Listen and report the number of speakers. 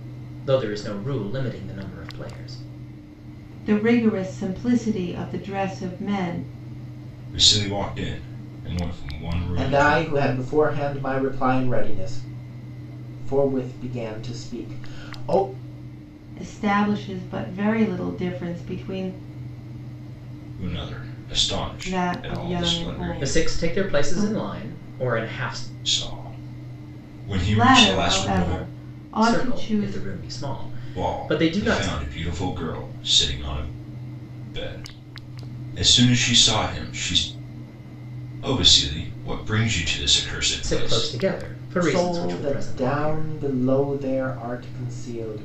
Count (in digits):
4